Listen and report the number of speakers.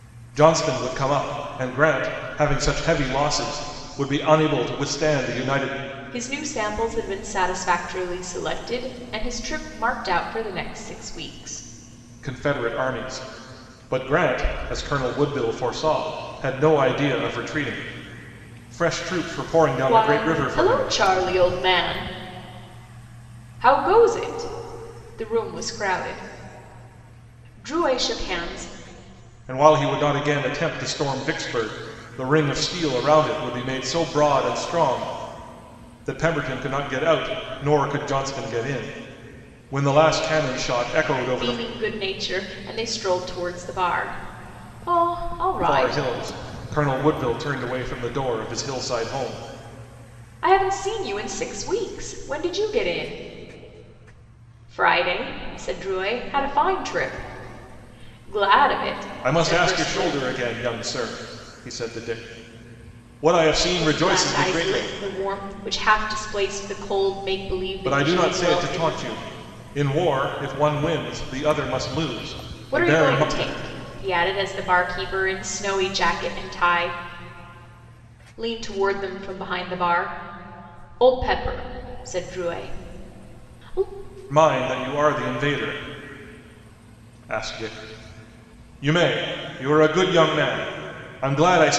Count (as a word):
two